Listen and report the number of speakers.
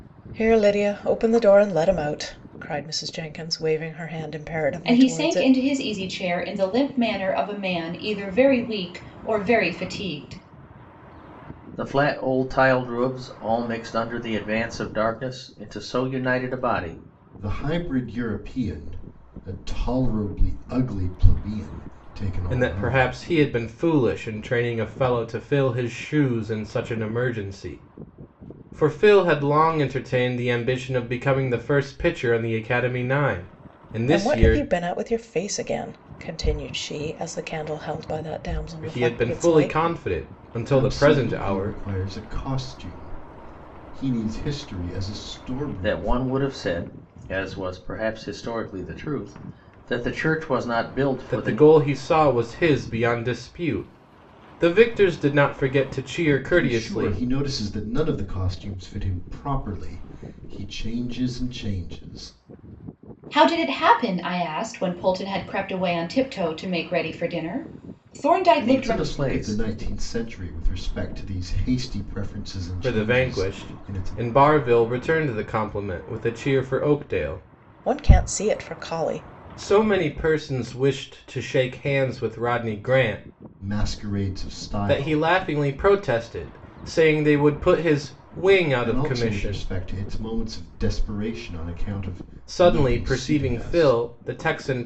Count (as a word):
five